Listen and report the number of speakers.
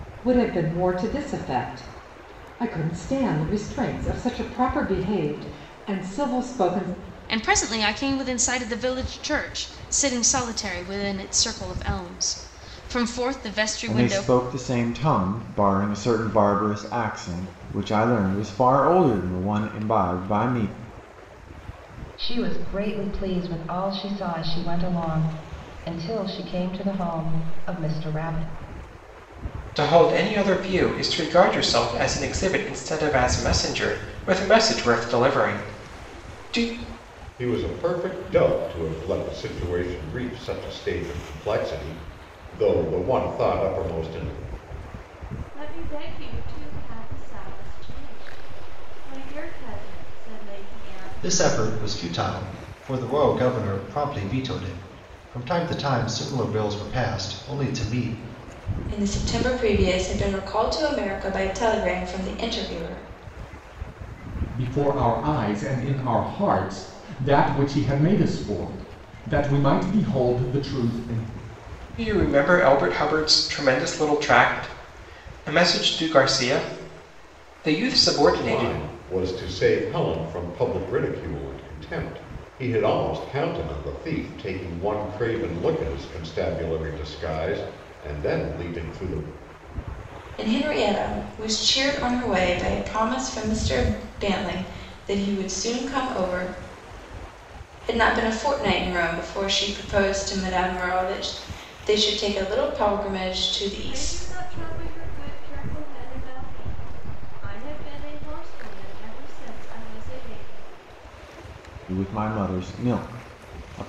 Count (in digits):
10